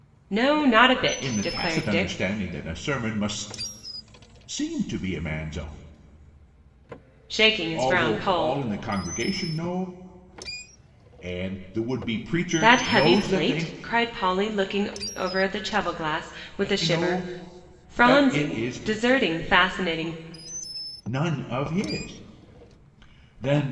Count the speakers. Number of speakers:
2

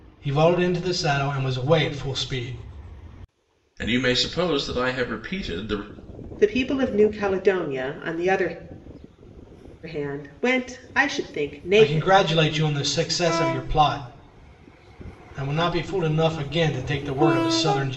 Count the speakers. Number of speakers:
3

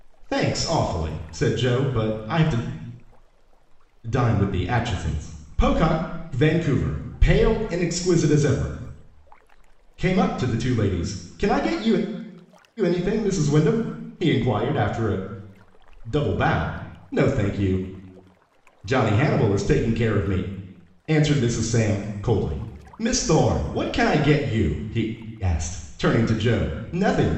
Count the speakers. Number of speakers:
1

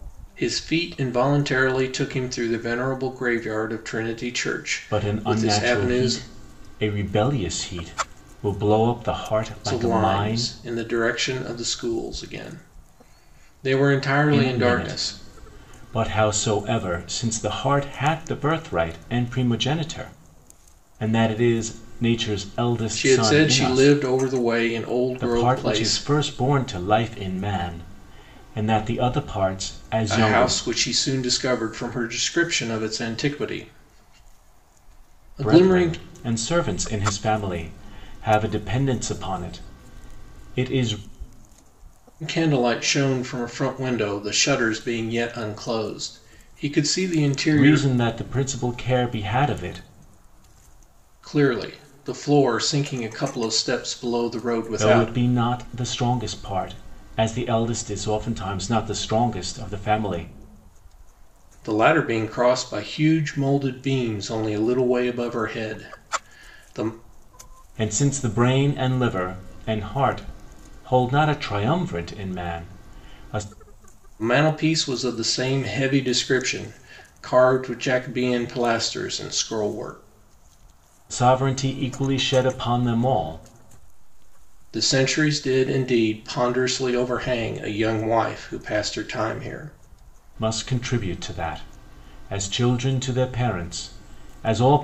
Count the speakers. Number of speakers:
2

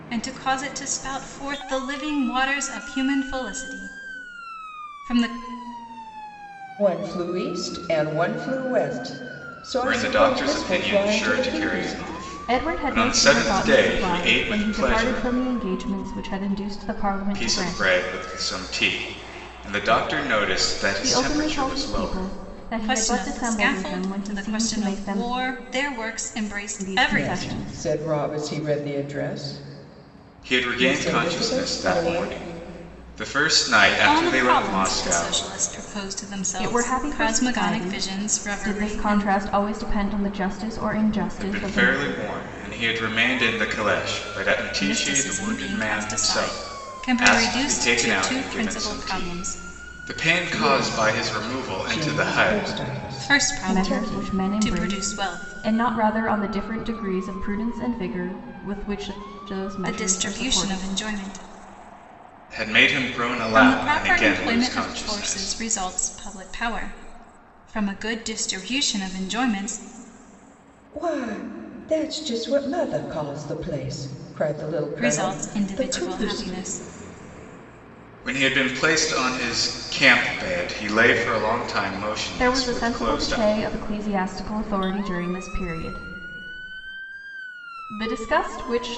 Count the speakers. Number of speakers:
4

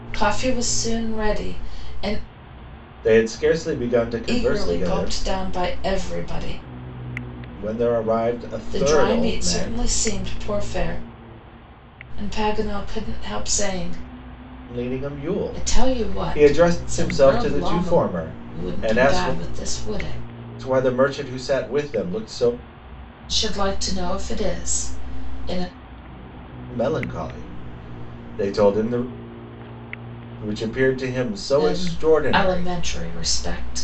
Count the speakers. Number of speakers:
2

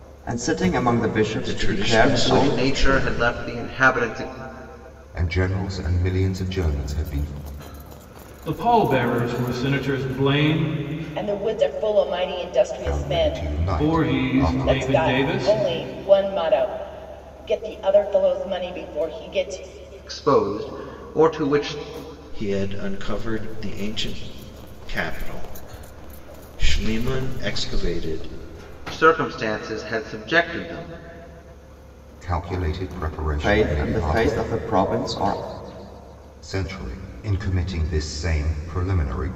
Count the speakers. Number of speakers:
6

